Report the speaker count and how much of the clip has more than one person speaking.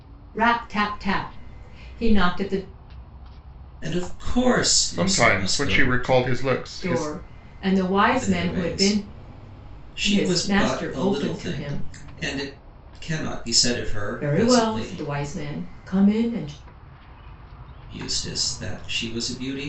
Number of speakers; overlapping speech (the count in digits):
3, about 27%